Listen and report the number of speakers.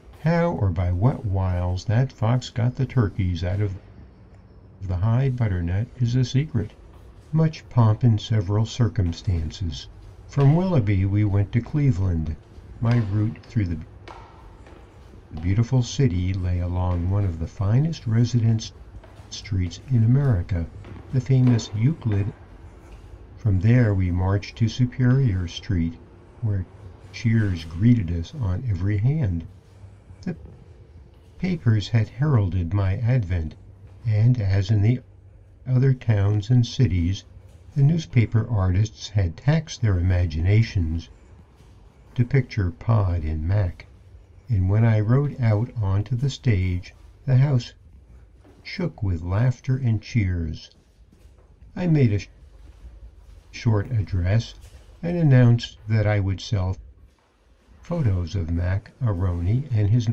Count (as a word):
one